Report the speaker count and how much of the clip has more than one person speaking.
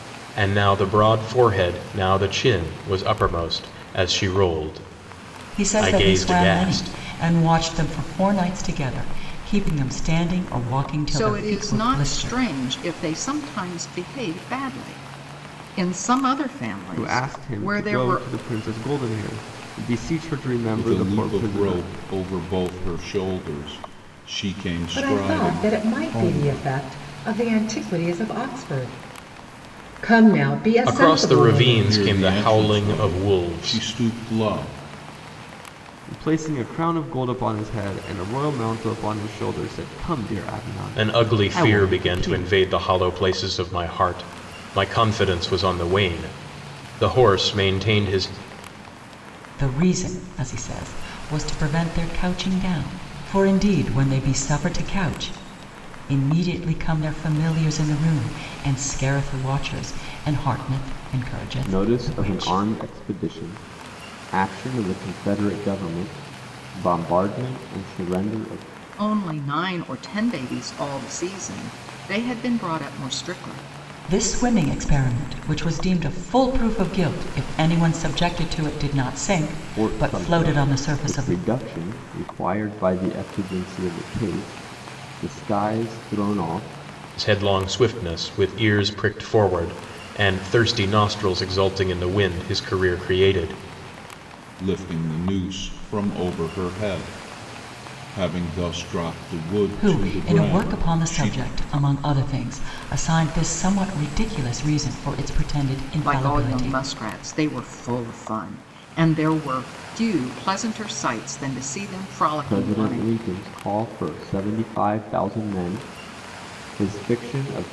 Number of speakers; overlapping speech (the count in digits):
6, about 15%